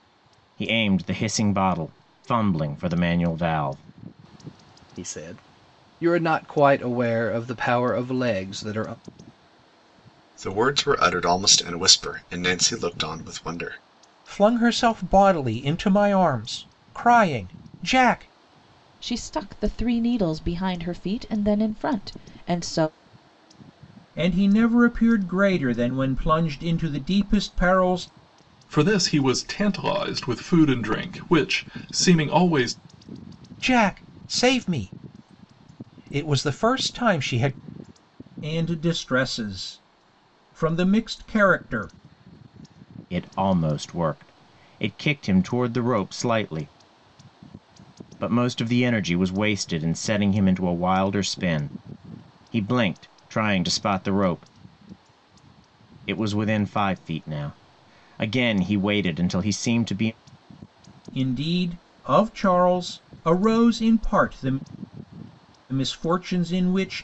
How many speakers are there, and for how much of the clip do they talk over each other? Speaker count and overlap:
seven, no overlap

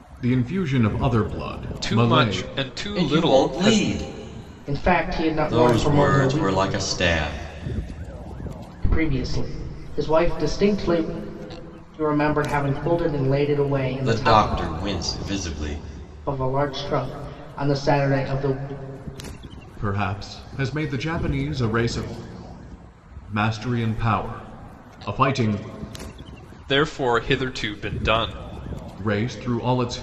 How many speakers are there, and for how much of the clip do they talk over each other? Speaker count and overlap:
four, about 11%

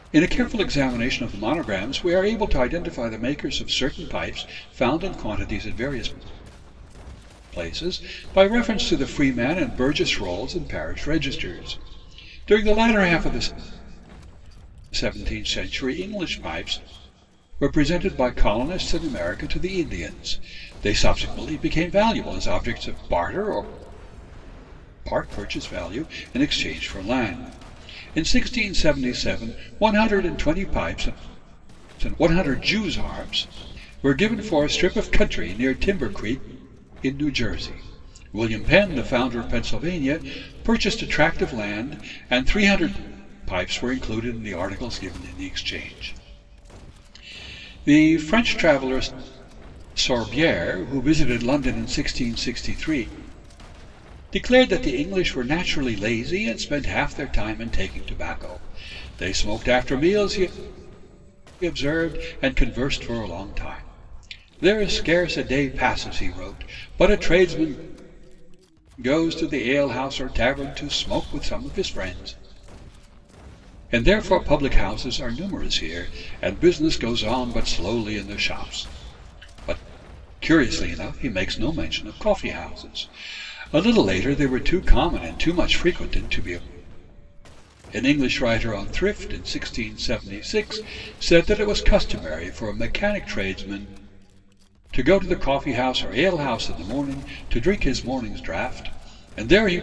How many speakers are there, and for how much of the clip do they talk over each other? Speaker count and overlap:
one, no overlap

